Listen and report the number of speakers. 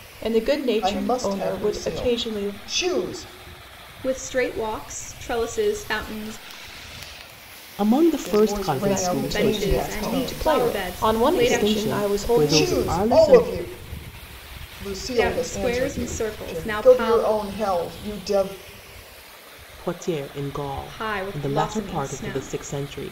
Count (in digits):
4